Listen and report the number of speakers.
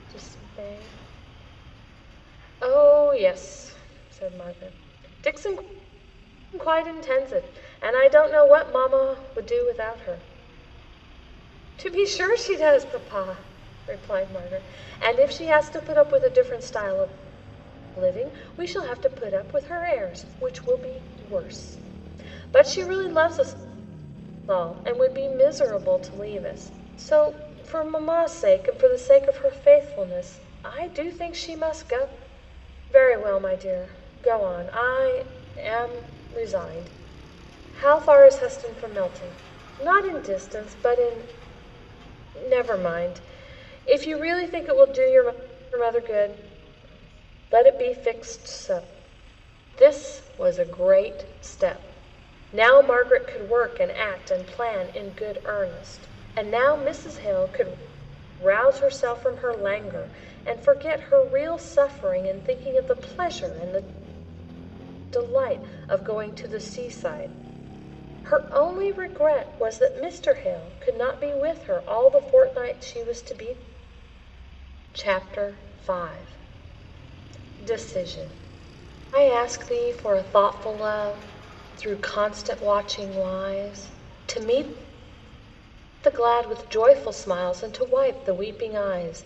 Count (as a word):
one